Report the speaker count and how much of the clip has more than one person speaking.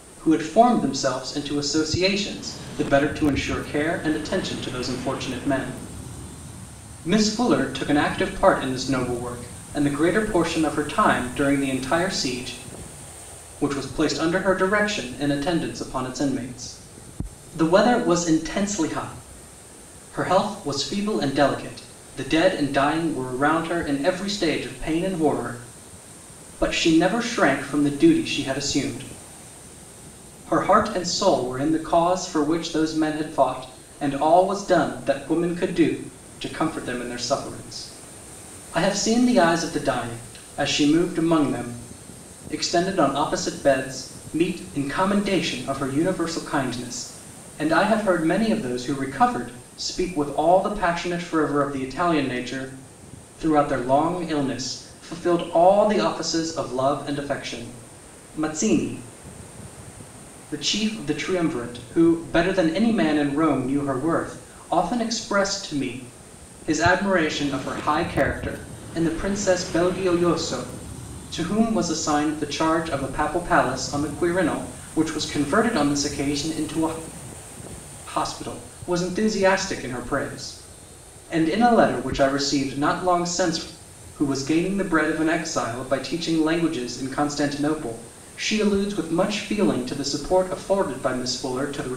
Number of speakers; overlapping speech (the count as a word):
one, no overlap